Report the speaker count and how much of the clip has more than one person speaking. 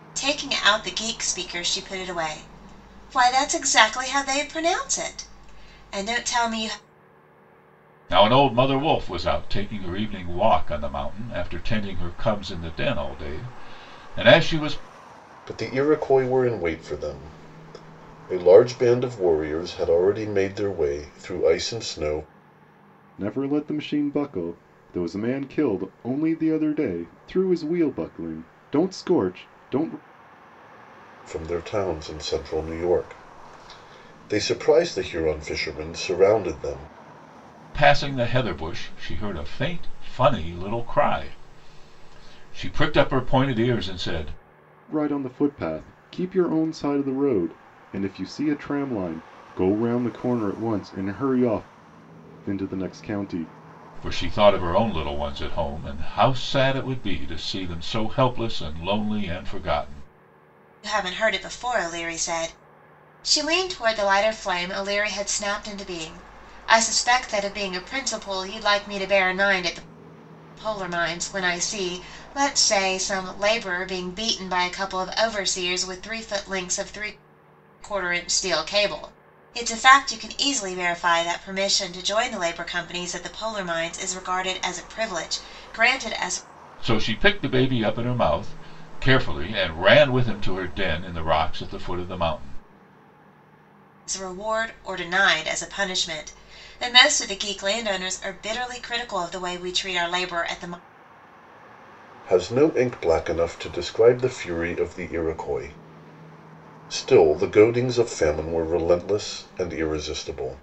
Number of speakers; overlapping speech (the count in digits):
4, no overlap